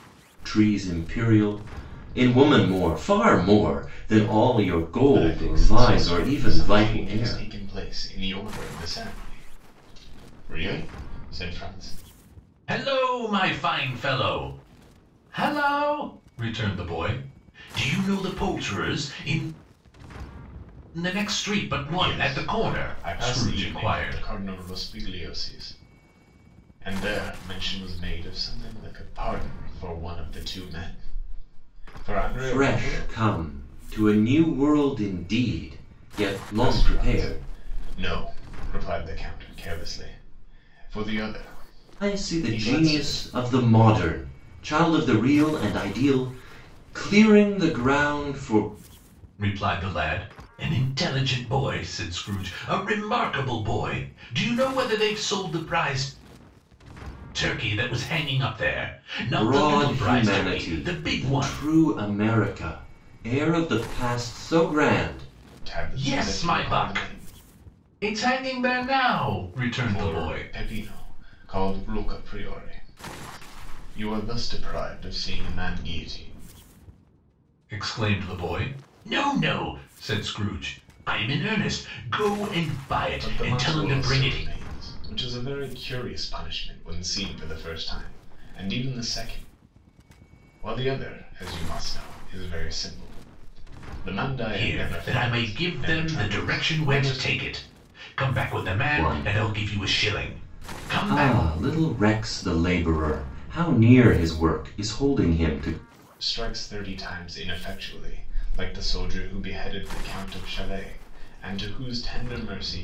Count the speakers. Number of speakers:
three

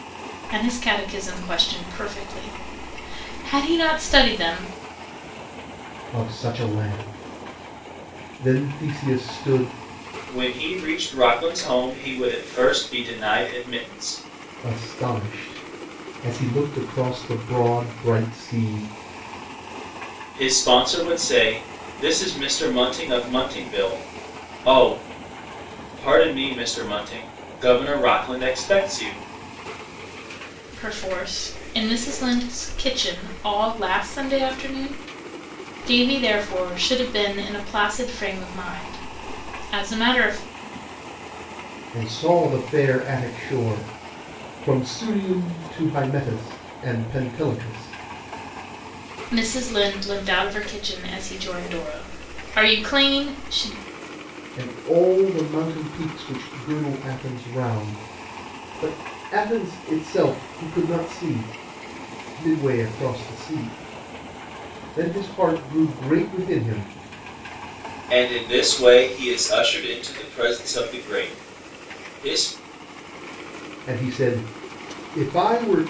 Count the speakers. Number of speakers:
three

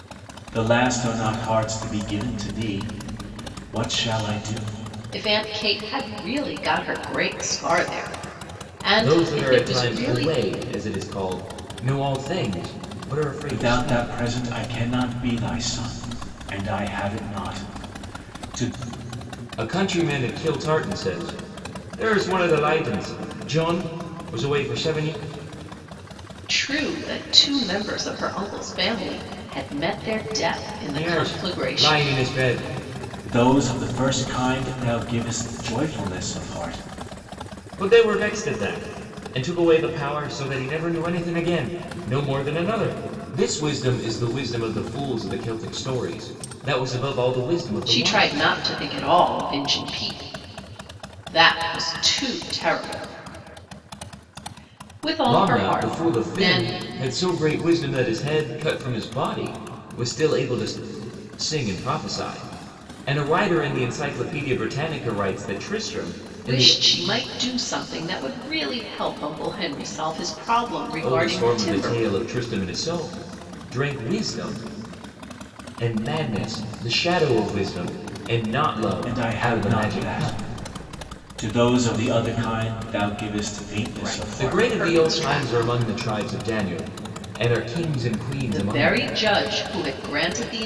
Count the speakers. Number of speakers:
three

